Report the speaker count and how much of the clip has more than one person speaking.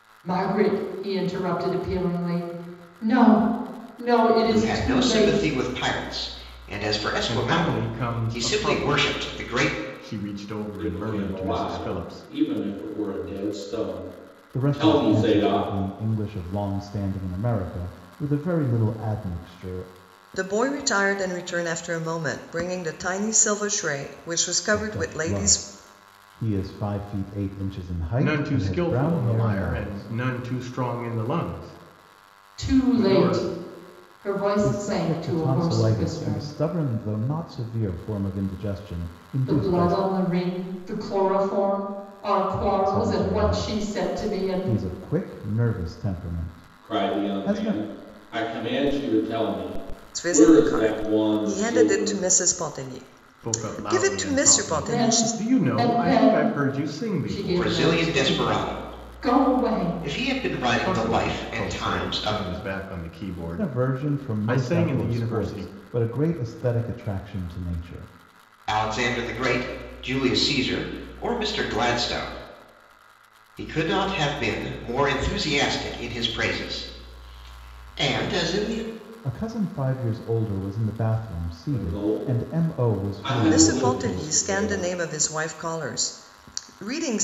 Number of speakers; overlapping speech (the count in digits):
6, about 36%